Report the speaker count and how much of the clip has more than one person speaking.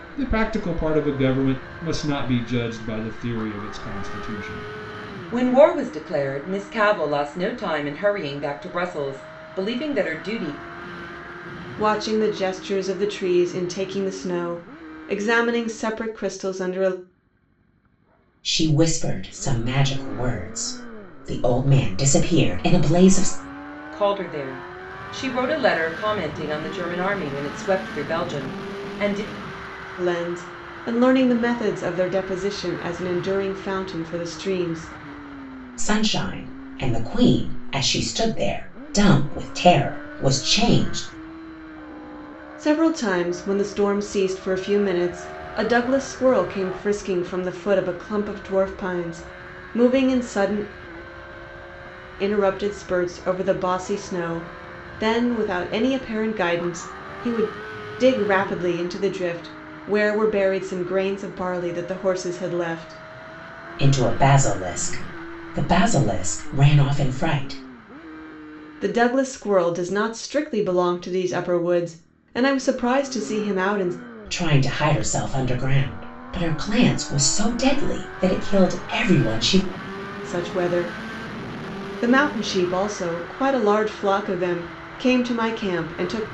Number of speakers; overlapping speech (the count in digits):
4, no overlap